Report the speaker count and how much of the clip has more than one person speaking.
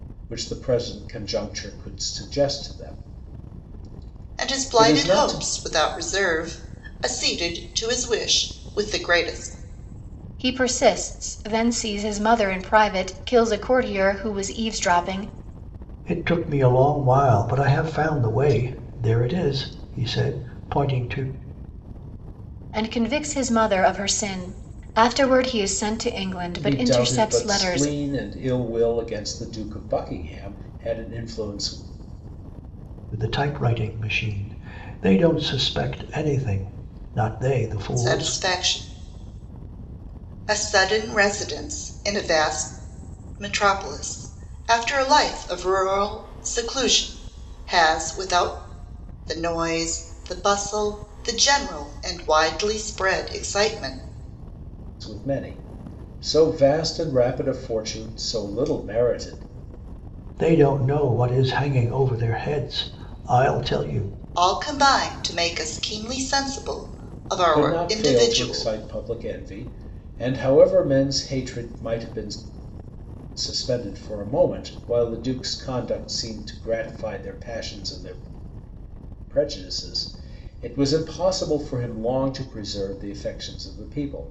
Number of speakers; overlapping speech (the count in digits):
4, about 5%